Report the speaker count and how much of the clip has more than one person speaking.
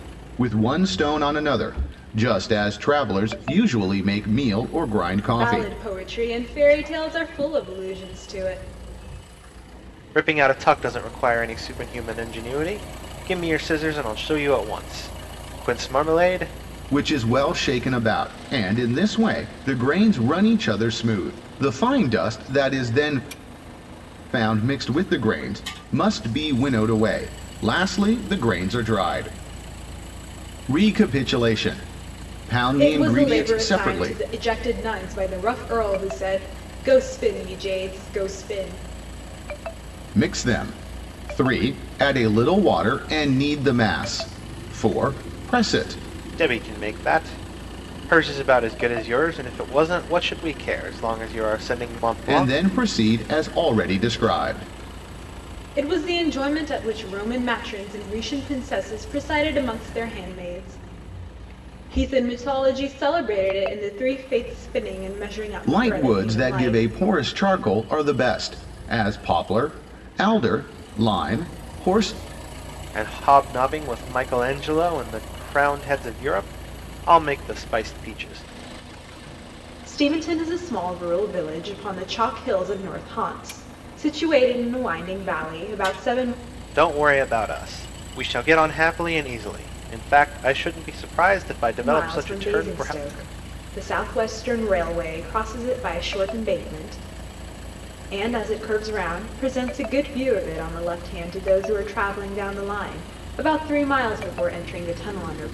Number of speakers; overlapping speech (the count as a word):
three, about 4%